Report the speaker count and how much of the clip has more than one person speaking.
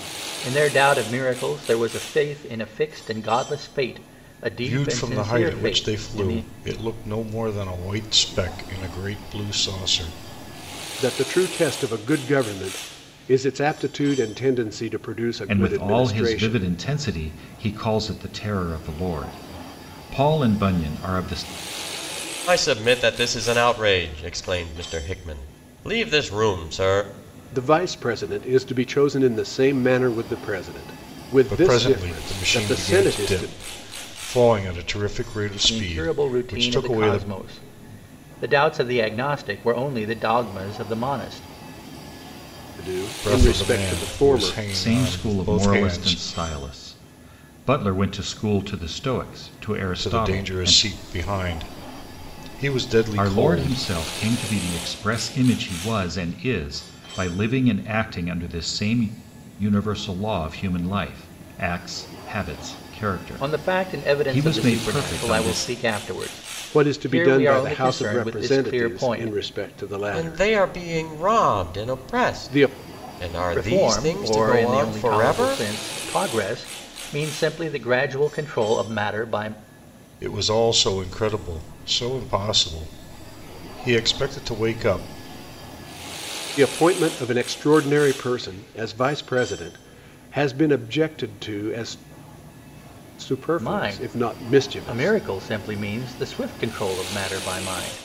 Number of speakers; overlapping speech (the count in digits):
5, about 23%